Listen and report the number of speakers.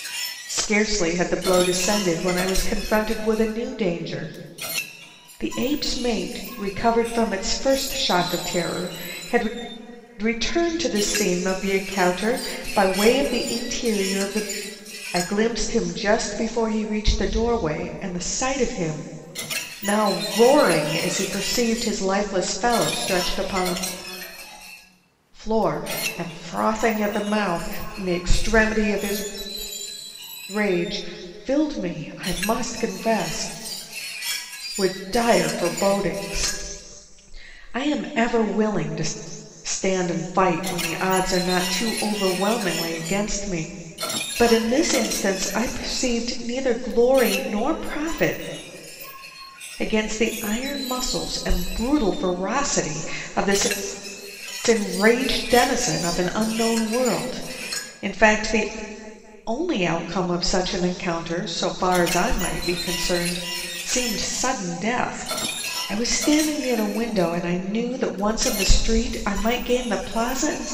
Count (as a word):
one